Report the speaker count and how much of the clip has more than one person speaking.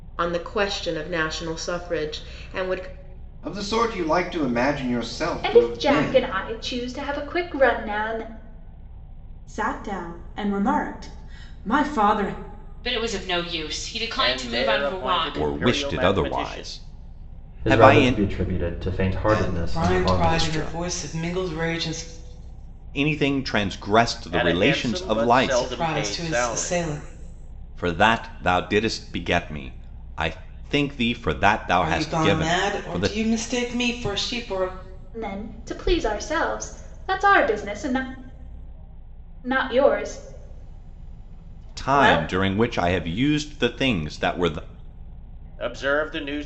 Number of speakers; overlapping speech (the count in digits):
10, about 22%